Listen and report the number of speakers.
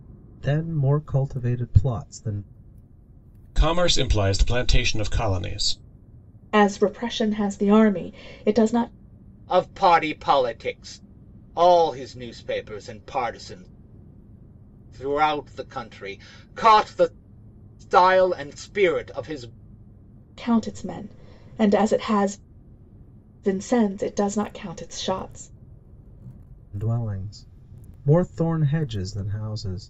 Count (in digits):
4